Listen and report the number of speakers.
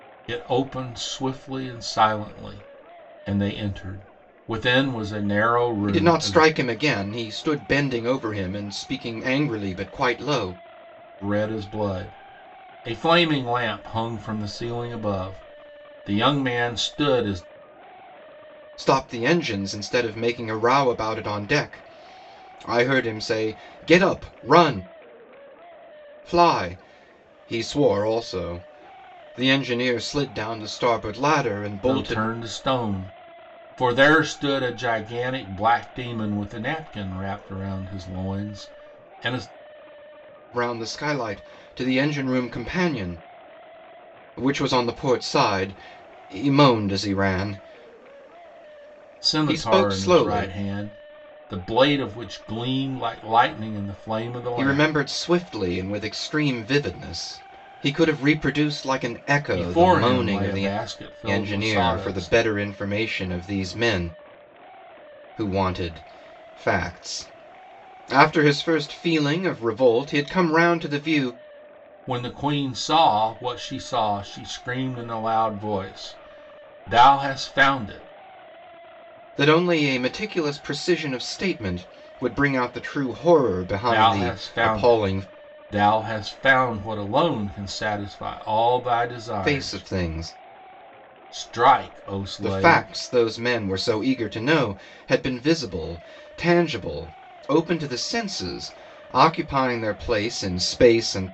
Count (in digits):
2